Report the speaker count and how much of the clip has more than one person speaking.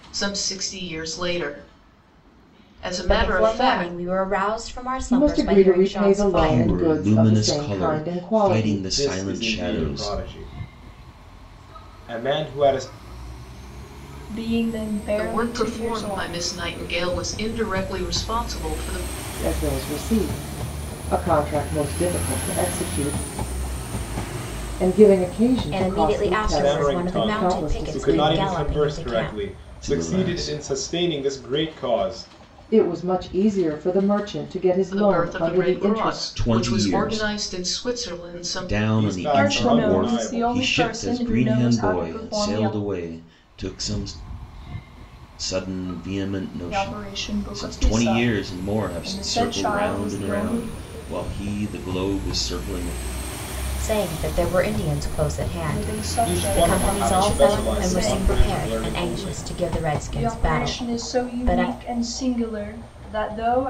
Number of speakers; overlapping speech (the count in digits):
6, about 46%